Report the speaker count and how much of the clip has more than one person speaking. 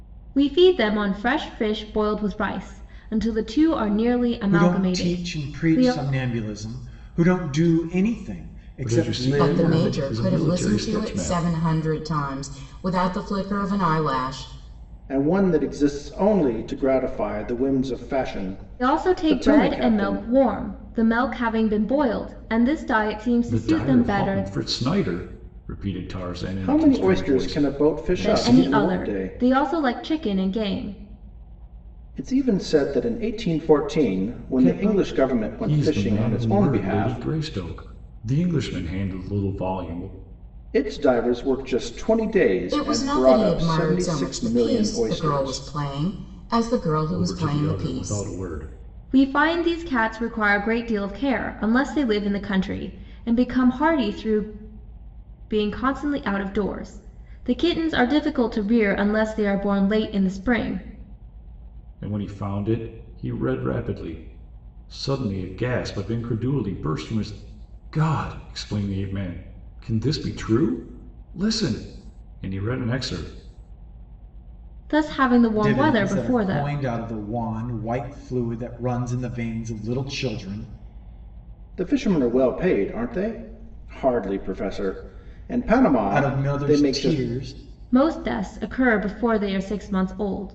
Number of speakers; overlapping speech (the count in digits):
5, about 21%